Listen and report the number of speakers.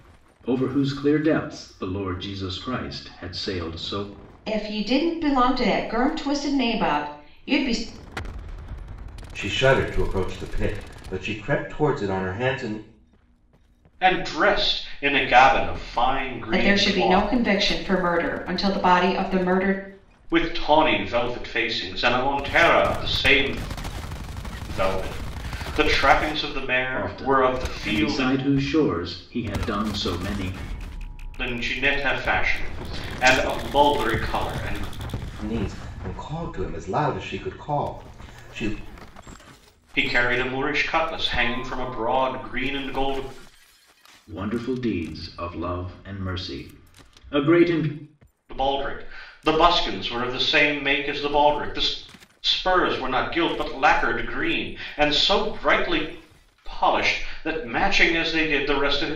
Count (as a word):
four